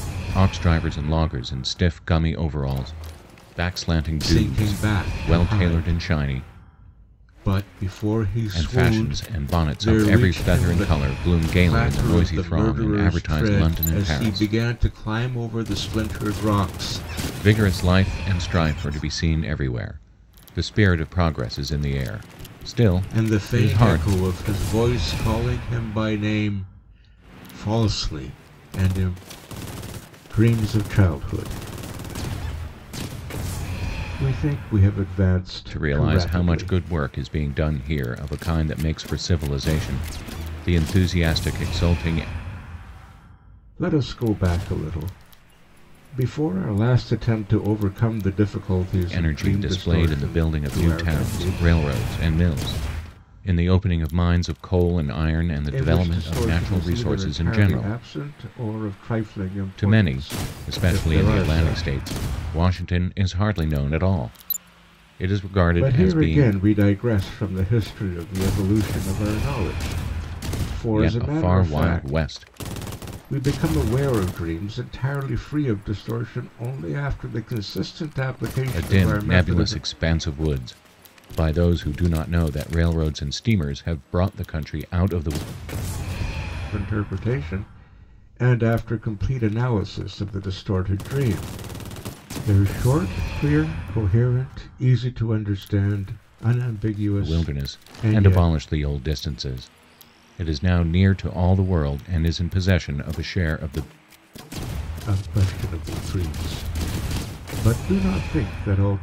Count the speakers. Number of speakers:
2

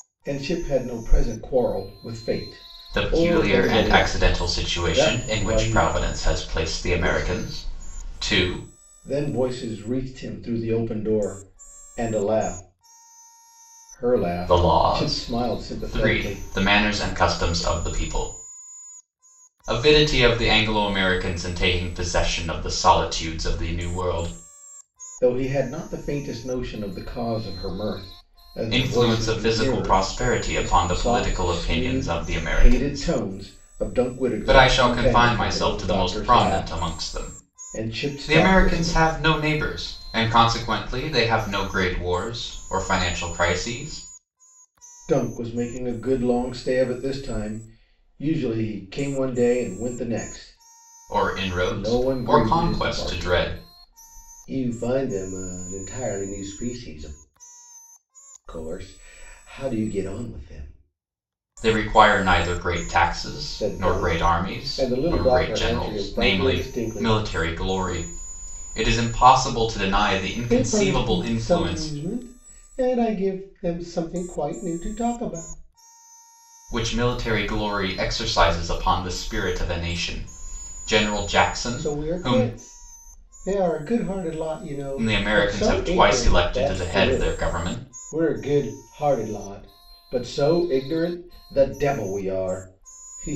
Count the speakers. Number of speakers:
2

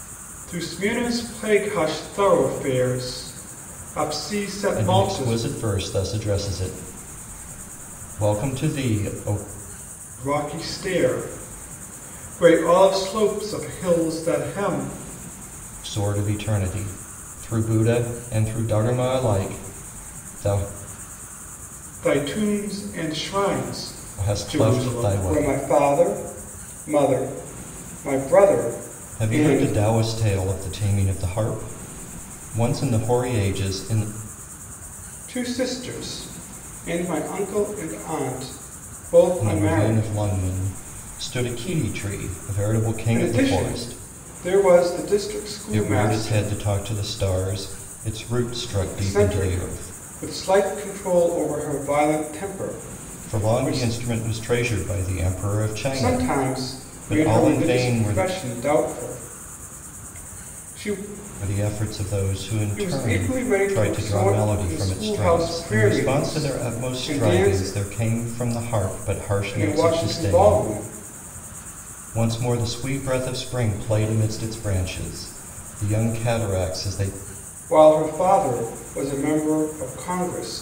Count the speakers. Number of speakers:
2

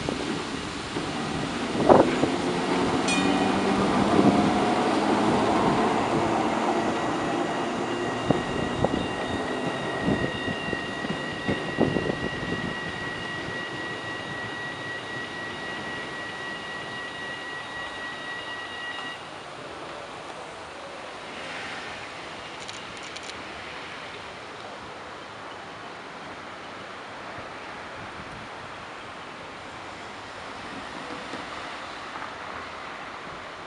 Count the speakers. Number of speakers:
0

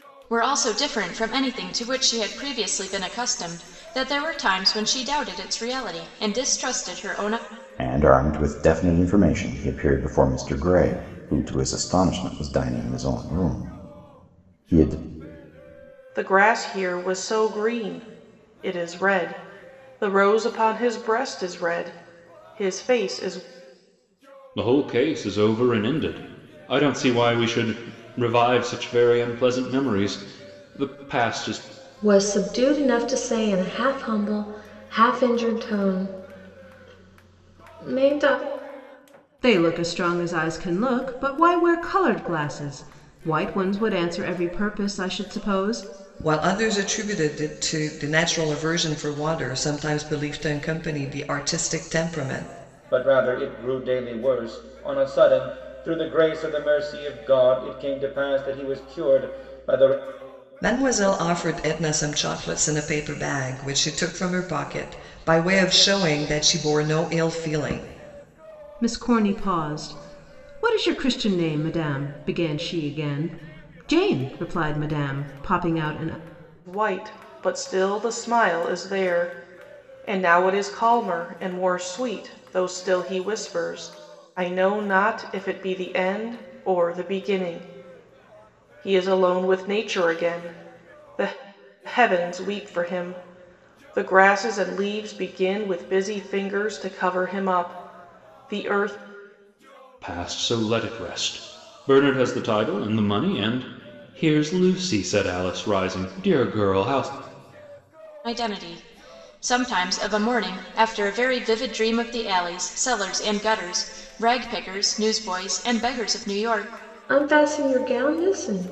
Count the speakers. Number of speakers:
8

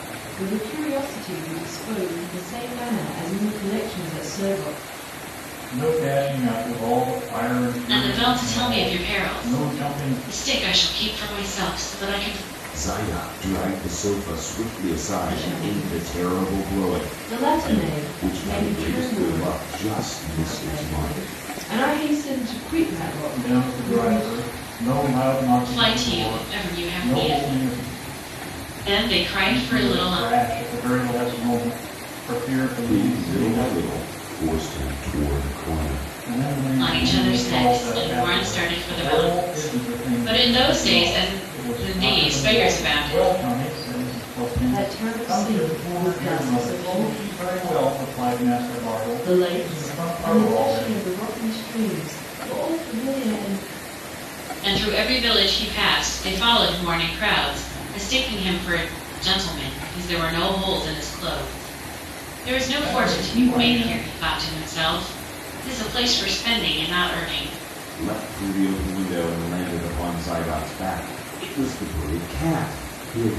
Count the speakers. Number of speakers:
4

